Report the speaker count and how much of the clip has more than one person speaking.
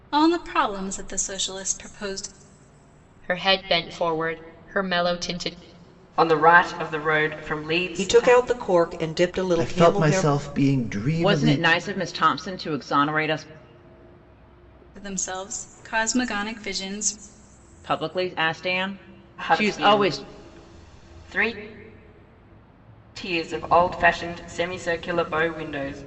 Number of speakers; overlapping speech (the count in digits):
6, about 10%